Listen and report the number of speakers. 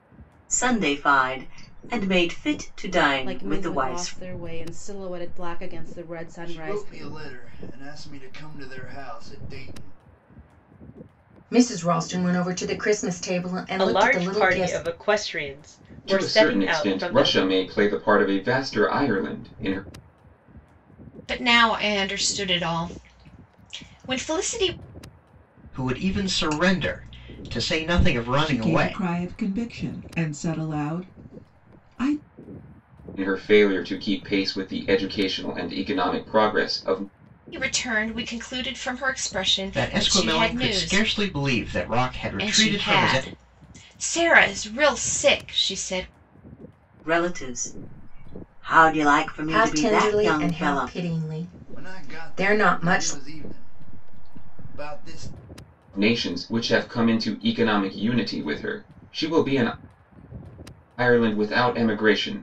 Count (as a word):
nine